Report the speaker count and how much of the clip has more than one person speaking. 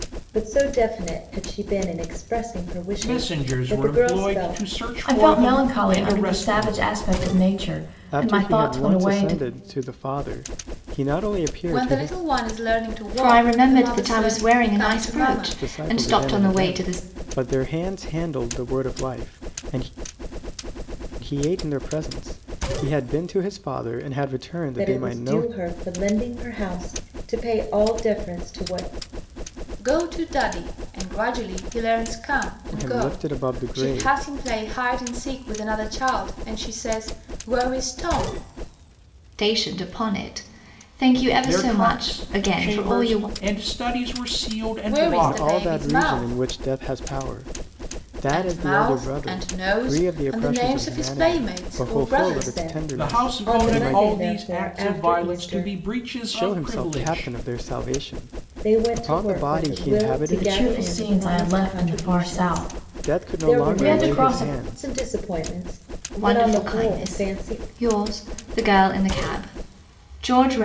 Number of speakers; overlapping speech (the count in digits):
6, about 44%